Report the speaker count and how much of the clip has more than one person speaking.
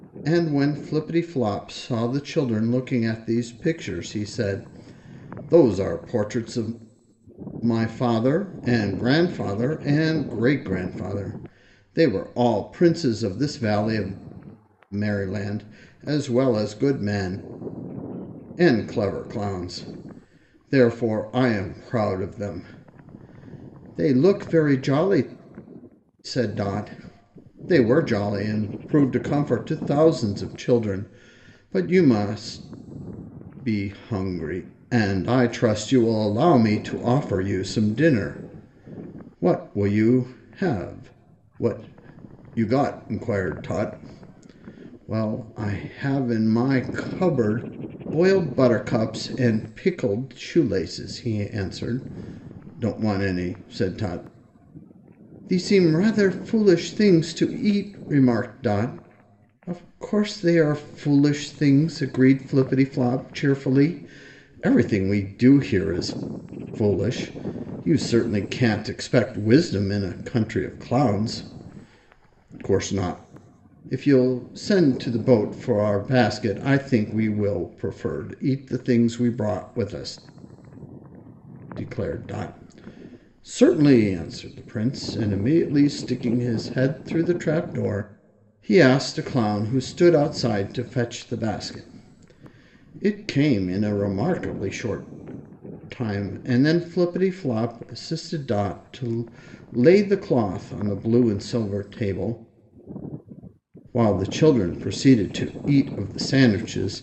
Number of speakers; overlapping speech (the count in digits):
1, no overlap